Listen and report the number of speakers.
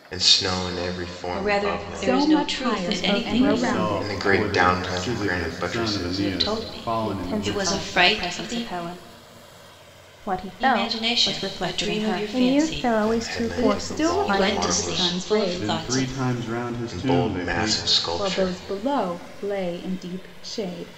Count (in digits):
5